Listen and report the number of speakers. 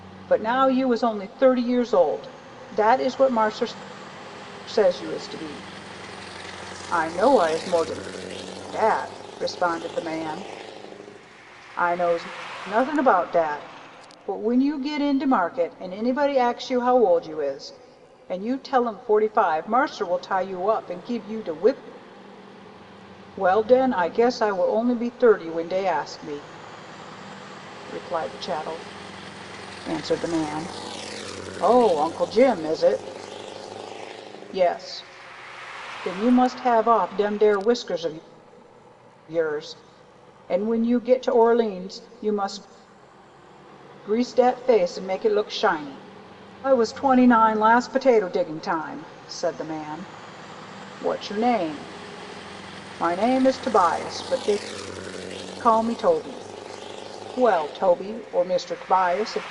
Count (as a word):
one